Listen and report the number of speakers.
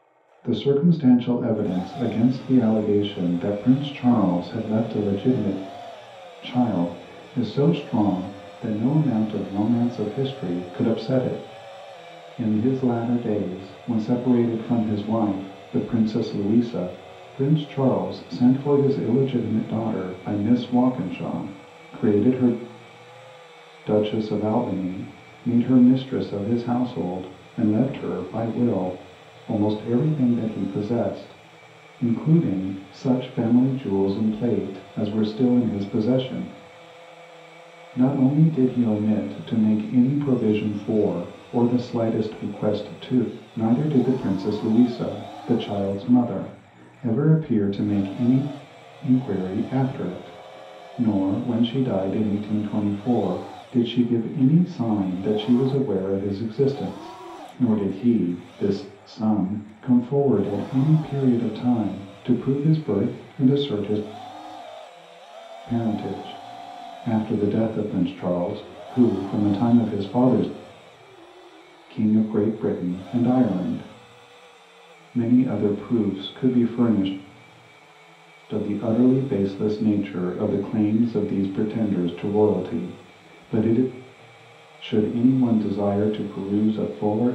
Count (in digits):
1